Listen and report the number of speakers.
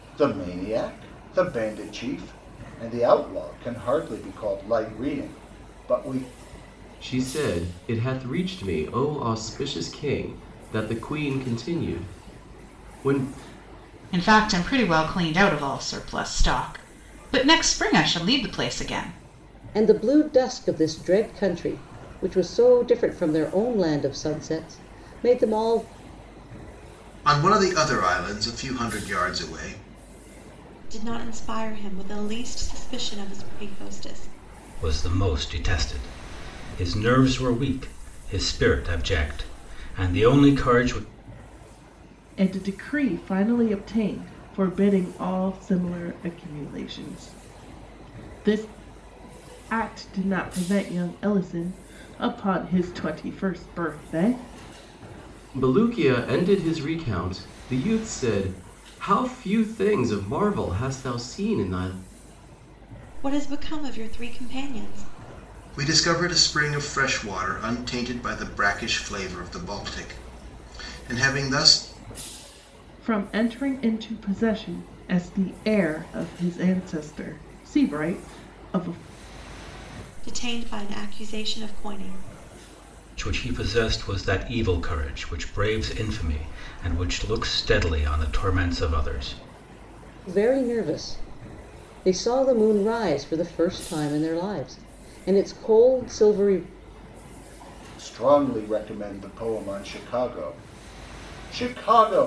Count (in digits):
8